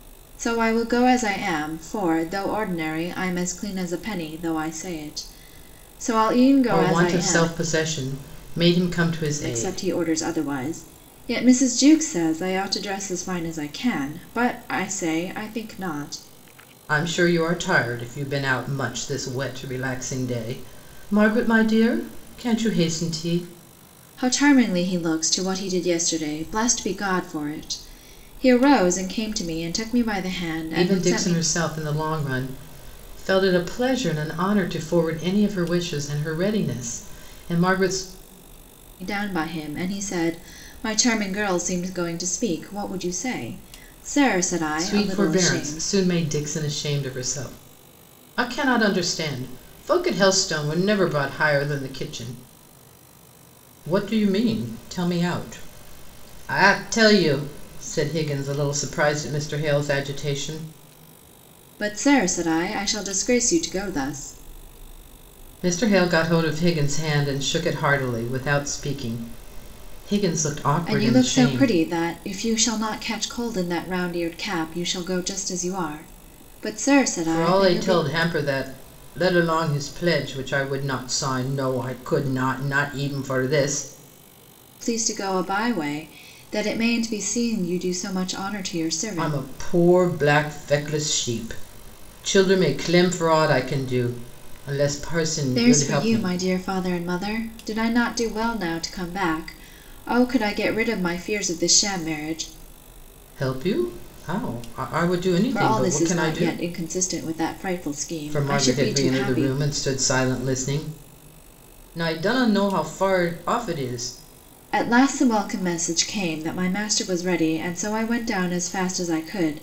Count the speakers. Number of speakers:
2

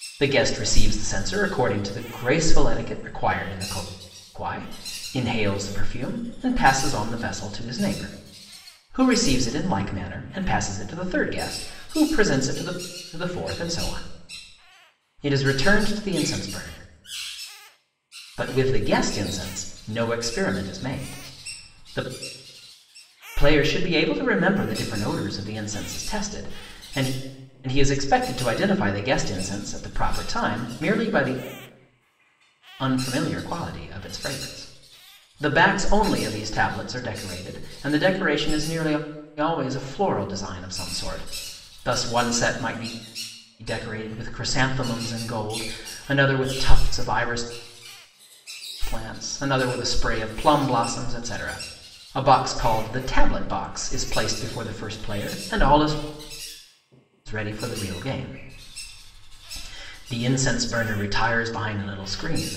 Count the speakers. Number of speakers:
1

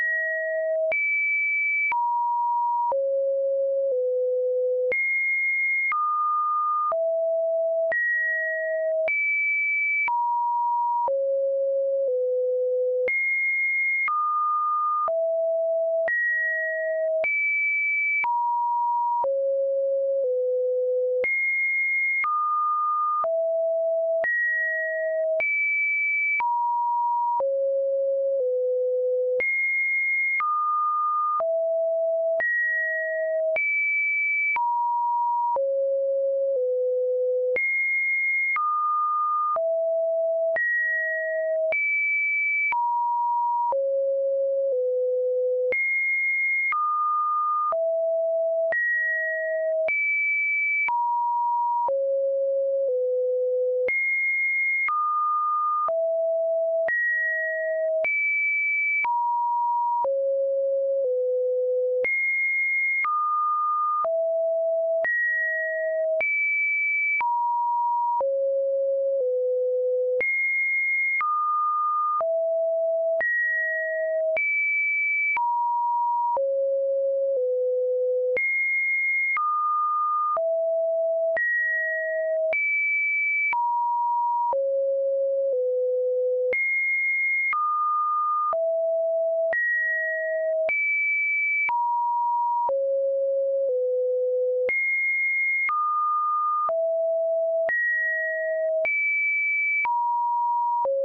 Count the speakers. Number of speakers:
0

